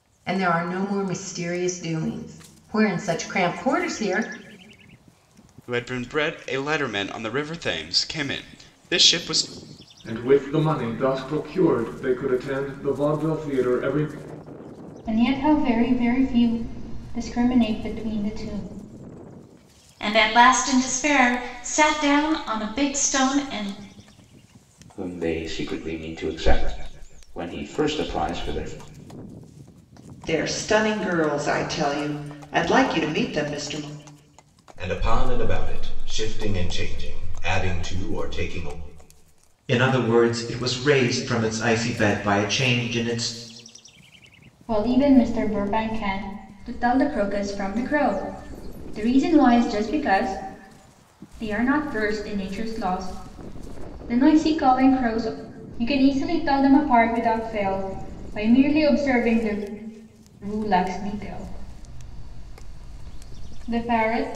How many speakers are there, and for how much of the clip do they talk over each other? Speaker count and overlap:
9, no overlap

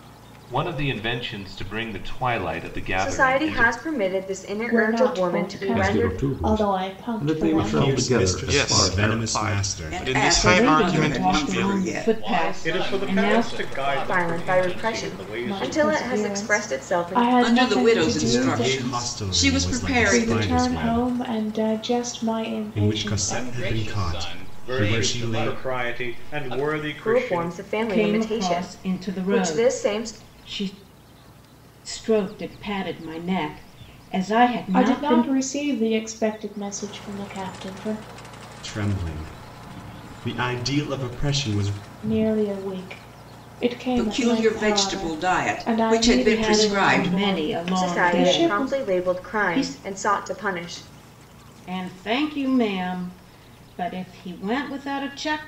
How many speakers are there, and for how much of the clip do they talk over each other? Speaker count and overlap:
10, about 54%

